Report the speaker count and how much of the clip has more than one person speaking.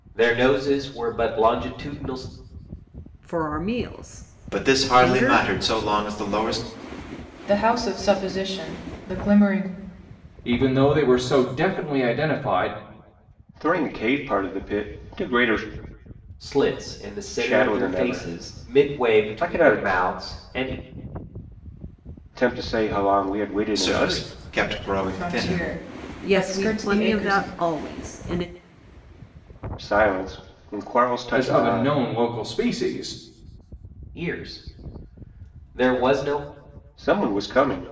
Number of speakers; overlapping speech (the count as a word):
six, about 17%